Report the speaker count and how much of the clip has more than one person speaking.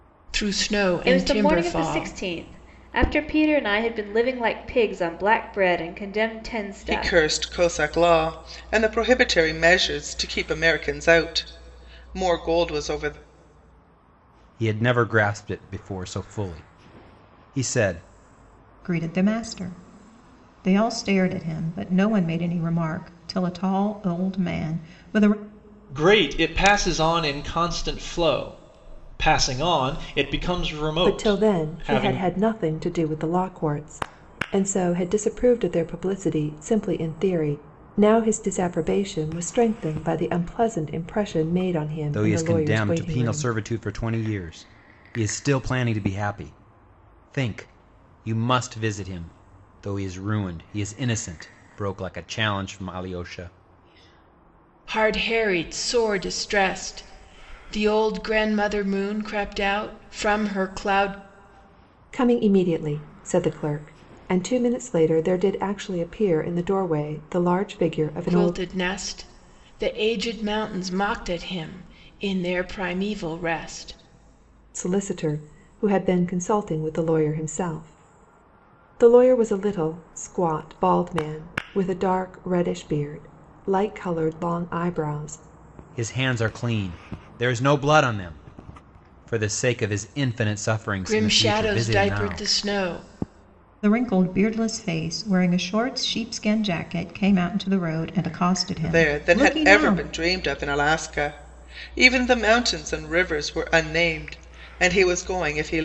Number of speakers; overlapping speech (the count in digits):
7, about 7%